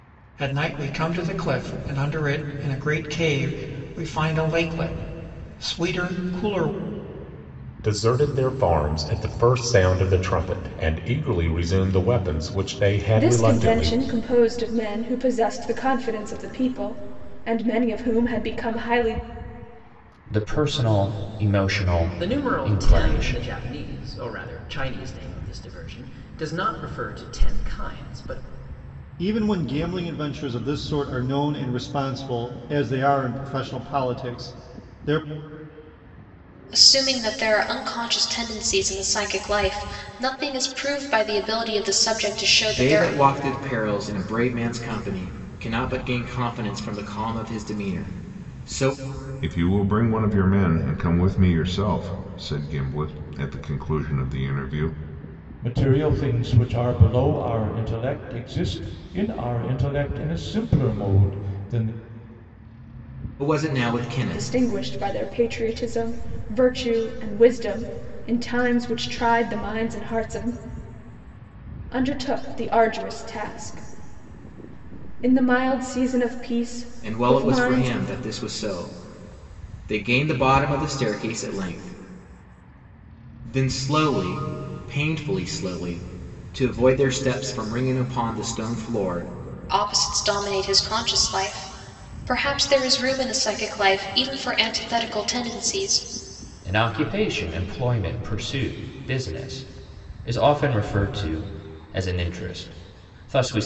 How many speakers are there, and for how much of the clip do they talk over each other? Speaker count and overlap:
ten, about 4%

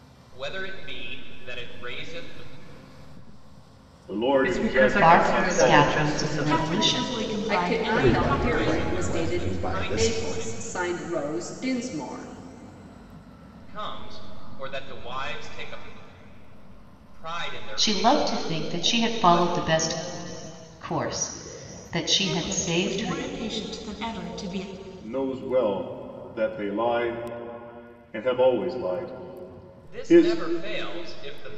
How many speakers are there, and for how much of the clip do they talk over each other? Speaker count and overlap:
seven, about 29%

